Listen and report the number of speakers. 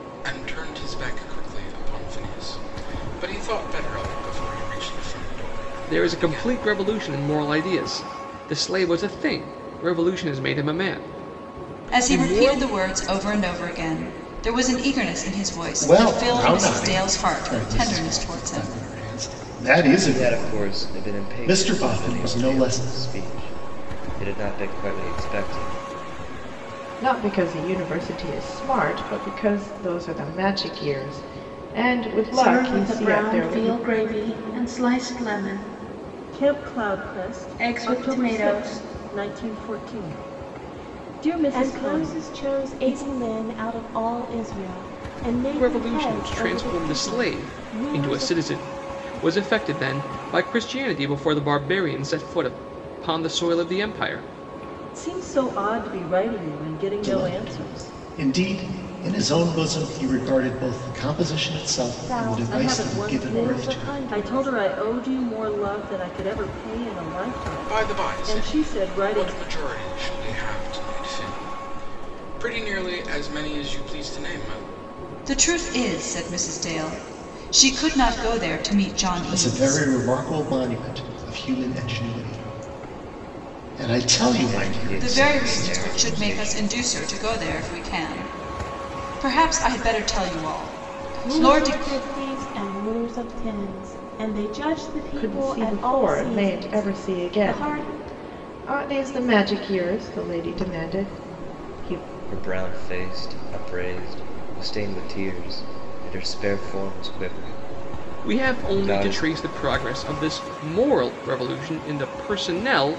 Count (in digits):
9